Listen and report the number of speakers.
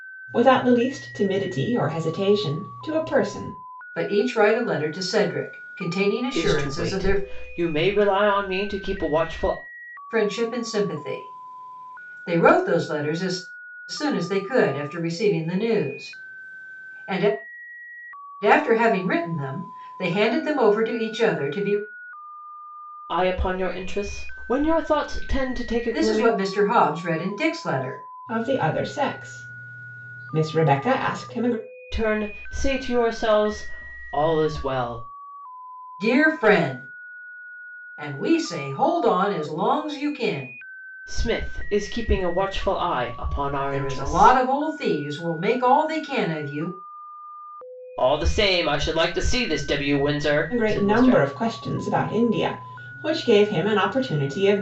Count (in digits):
3